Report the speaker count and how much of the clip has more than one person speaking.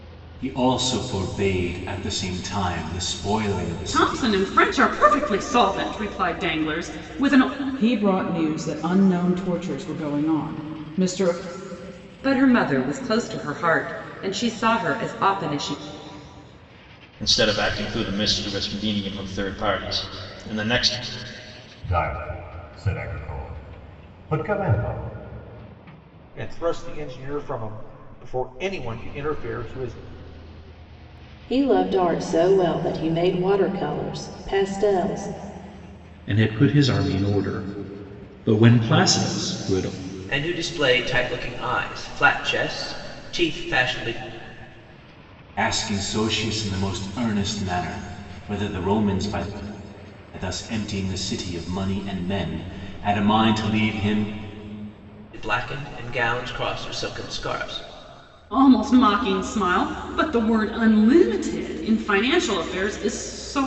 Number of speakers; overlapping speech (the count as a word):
ten, about 1%